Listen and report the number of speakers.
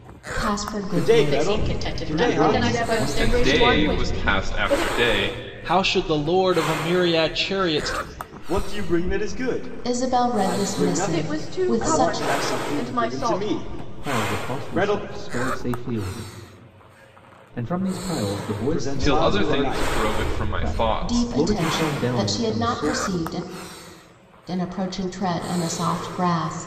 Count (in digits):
7